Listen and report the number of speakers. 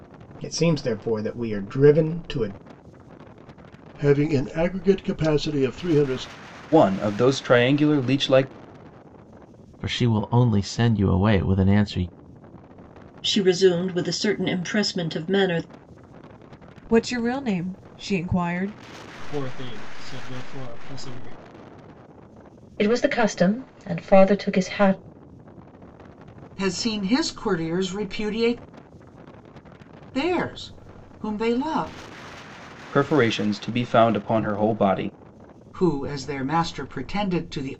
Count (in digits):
9